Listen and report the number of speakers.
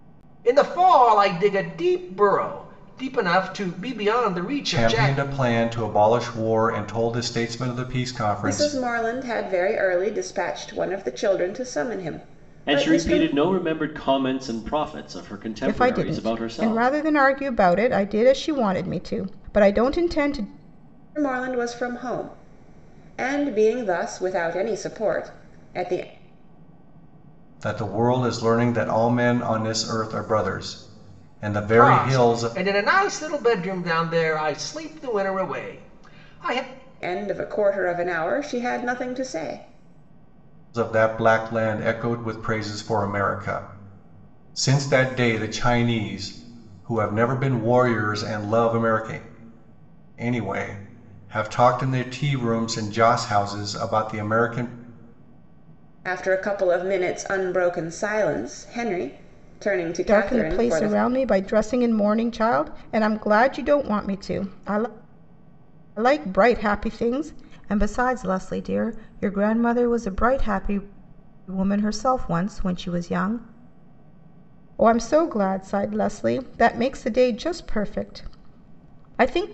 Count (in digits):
5